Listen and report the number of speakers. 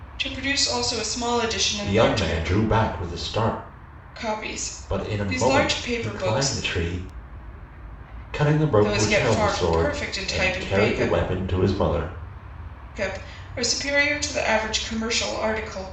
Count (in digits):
2